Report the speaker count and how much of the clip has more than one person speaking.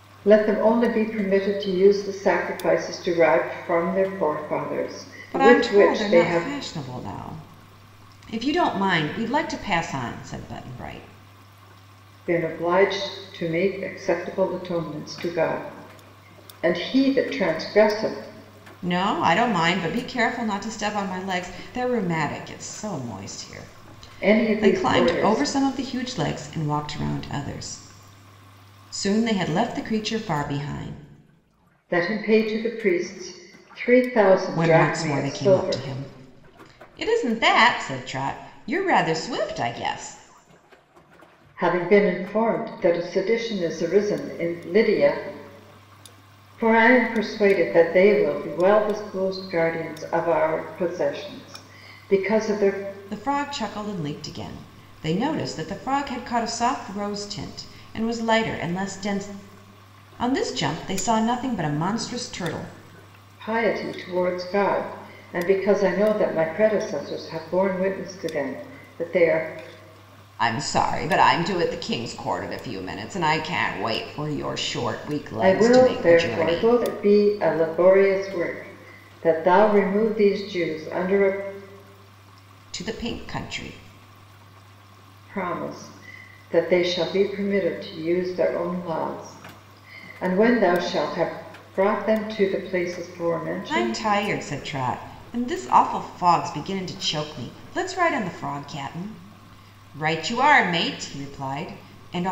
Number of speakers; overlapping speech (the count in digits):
2, about 5%